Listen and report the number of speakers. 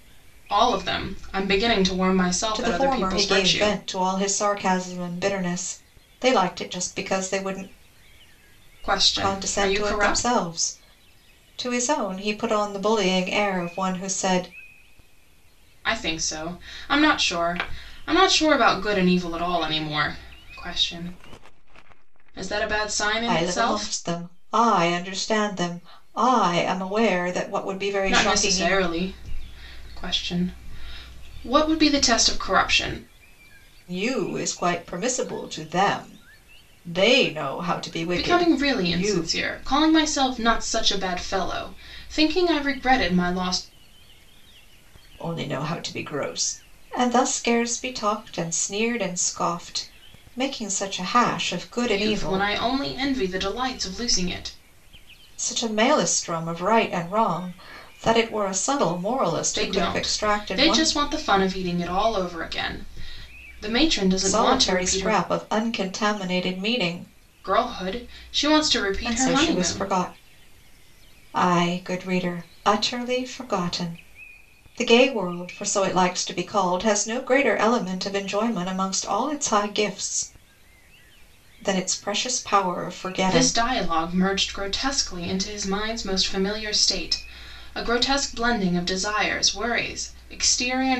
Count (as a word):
two